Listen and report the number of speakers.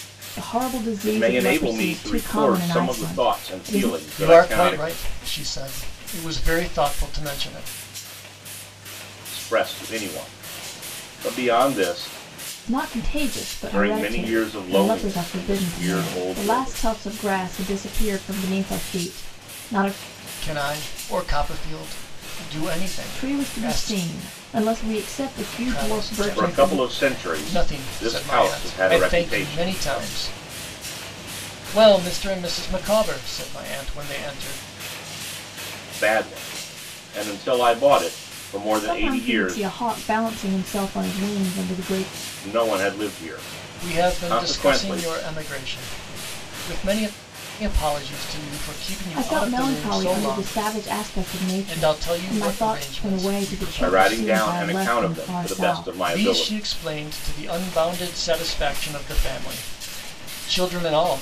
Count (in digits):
3